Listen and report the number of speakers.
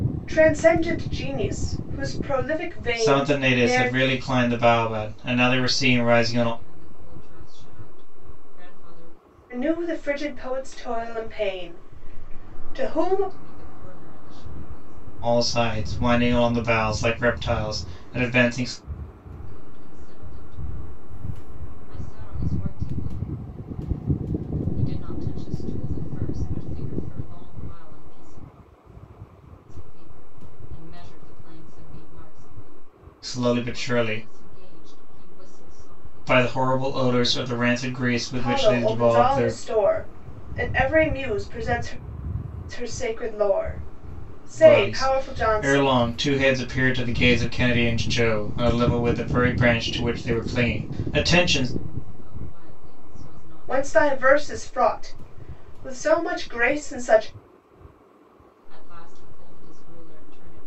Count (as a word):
three